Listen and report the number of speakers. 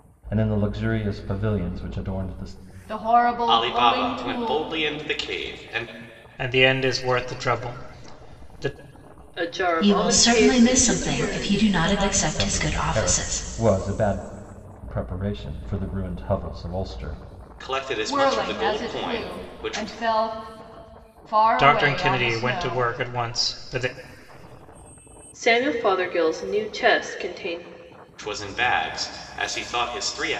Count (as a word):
six